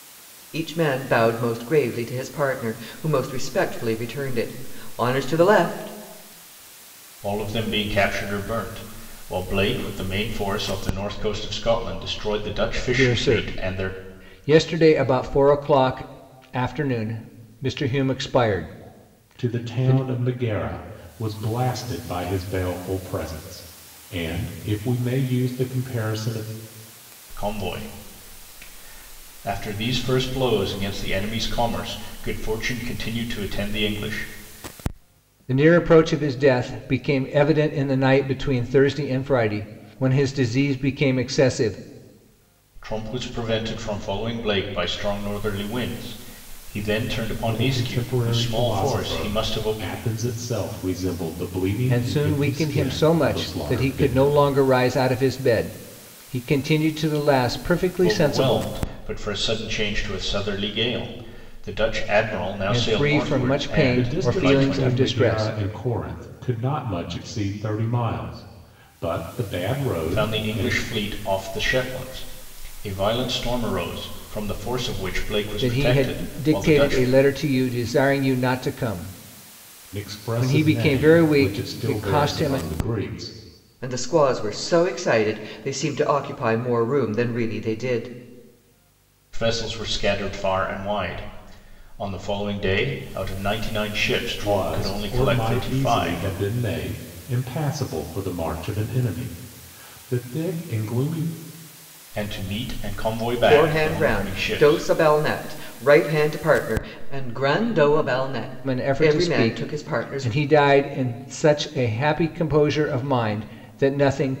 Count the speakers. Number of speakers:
4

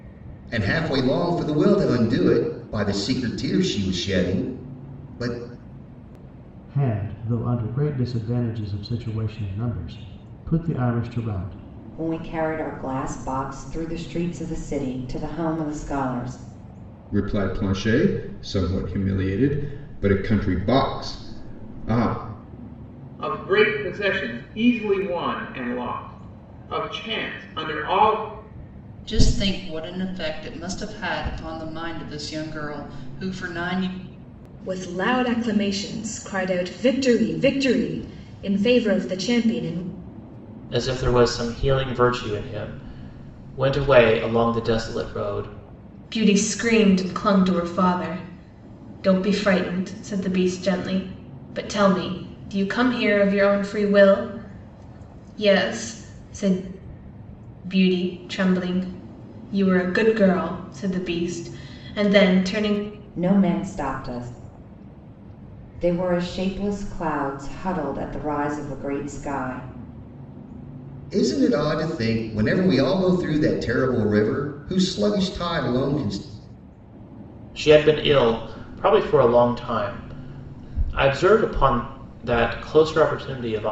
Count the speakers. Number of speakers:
9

